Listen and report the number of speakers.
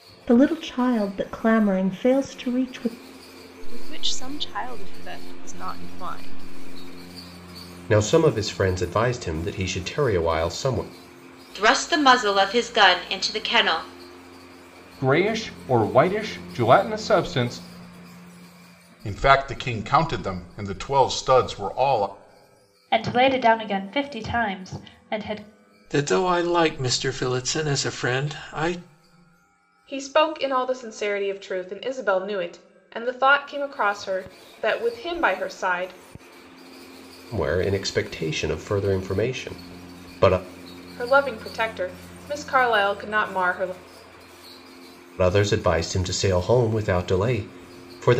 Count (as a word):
nine